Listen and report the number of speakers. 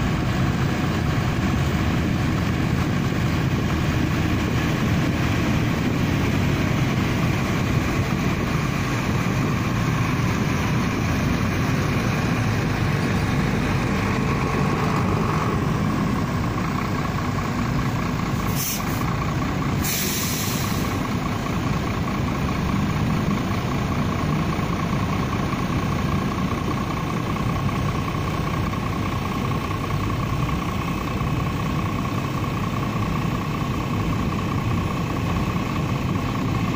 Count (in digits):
0